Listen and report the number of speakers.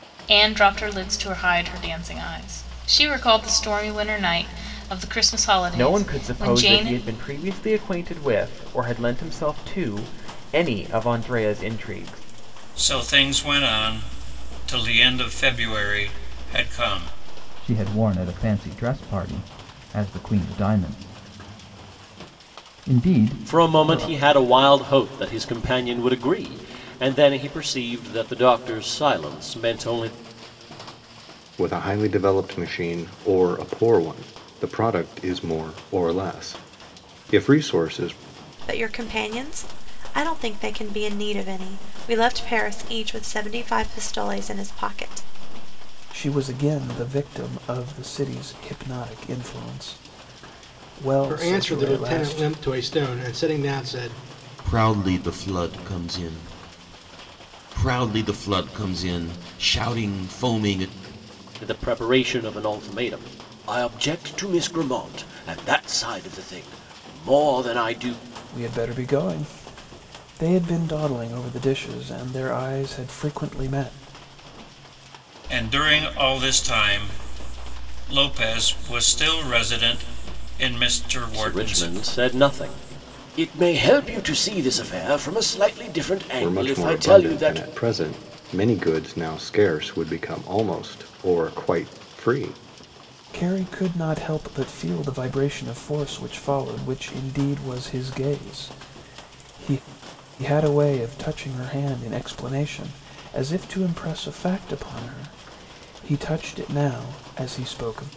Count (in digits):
10